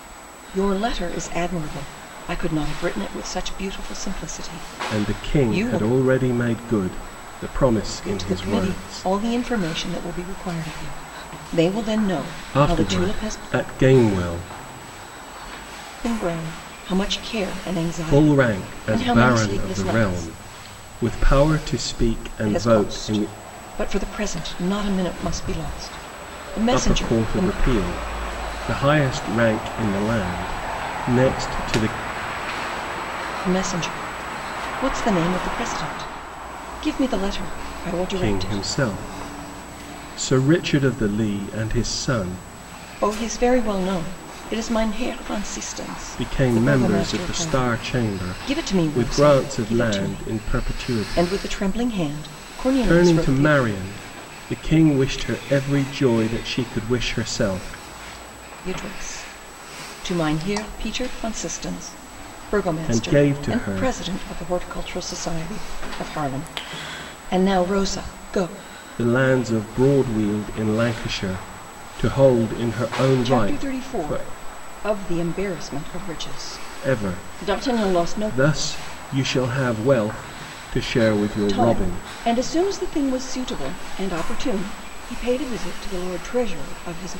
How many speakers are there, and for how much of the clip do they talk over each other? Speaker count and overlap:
2, about 20%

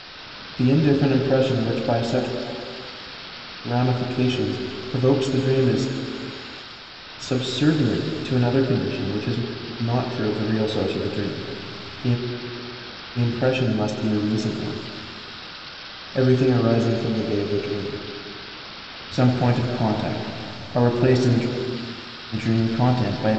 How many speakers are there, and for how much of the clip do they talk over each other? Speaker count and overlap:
1, no overlap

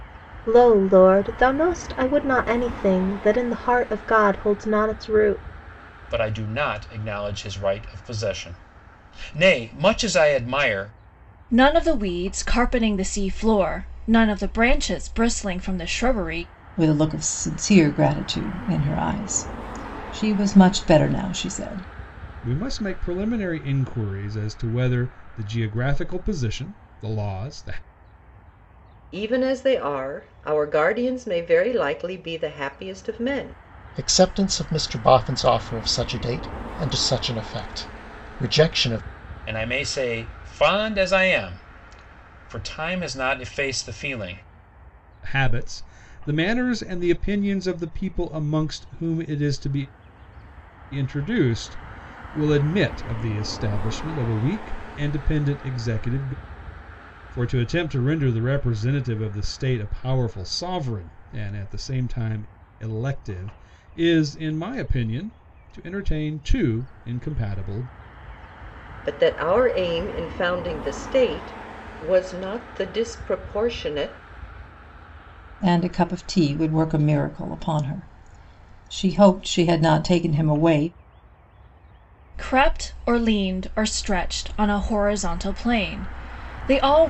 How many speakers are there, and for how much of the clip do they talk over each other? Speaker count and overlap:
7, no overlap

